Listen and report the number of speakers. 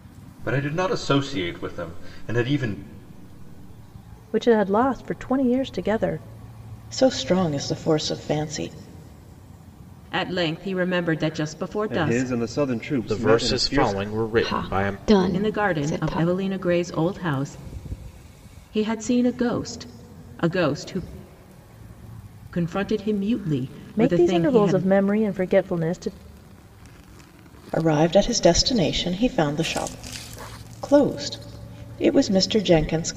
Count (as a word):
seven